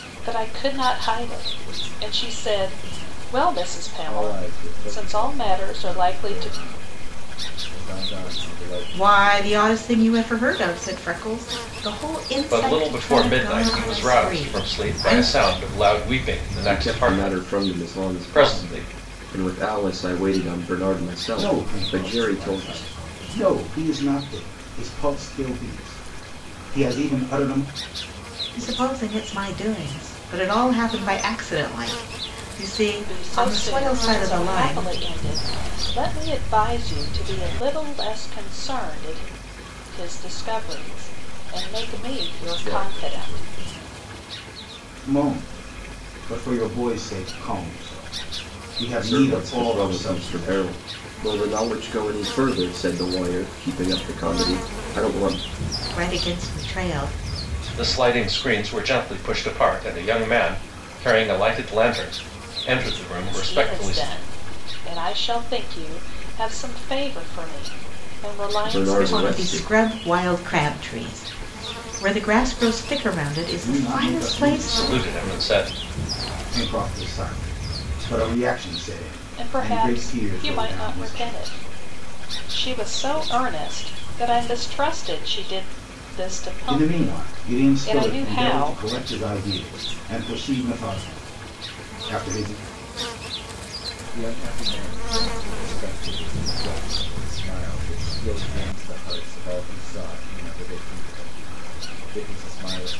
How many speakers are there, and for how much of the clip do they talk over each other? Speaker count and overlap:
6, about 22%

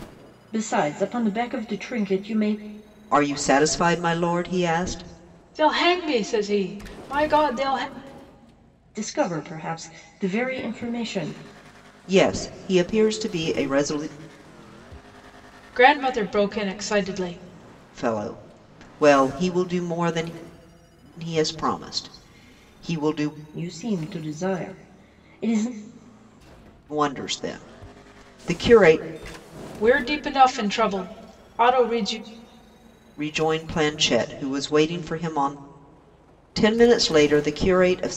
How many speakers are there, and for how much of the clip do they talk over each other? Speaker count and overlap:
3, no overlap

